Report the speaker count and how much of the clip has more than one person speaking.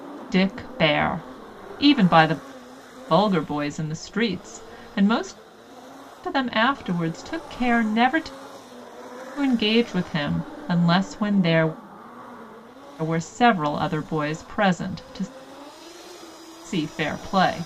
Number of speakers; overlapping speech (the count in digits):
1, no overlap